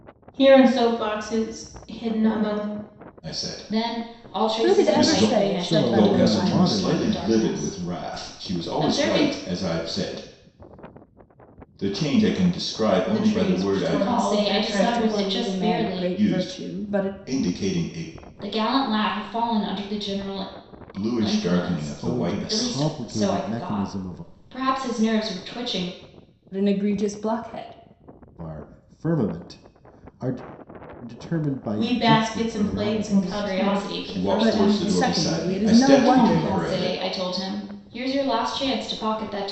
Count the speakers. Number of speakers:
five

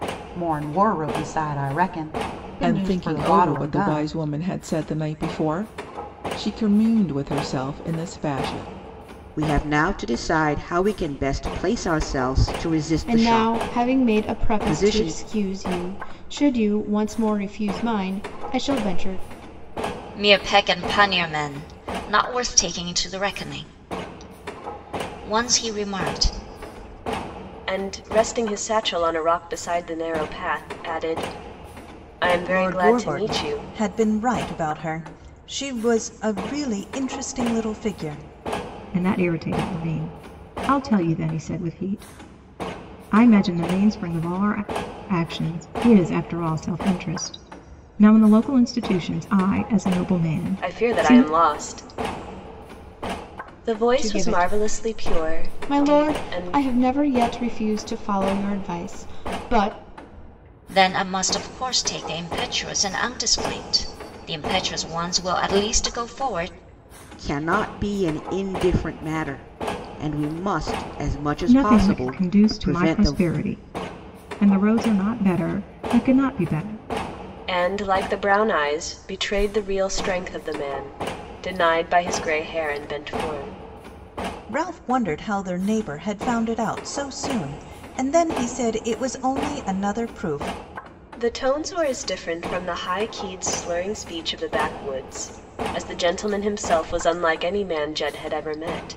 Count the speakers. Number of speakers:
eight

